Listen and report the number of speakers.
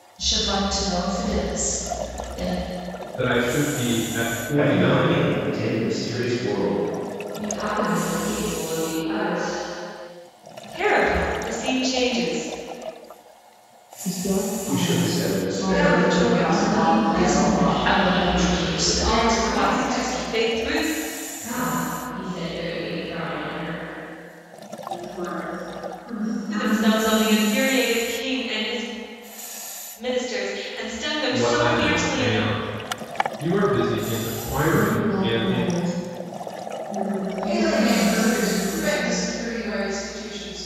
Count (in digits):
10